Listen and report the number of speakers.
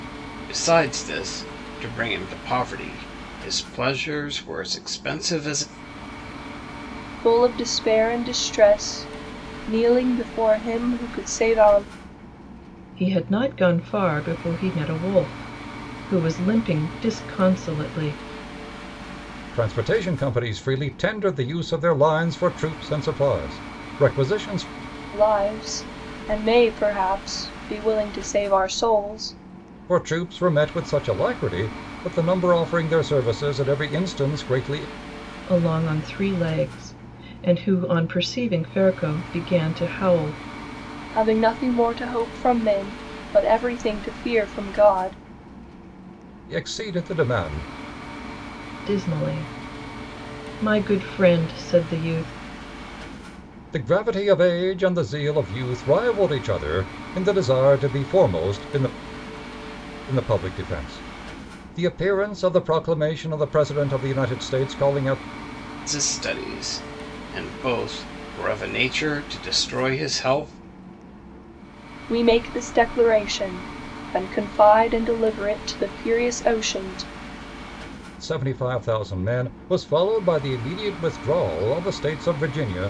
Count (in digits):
4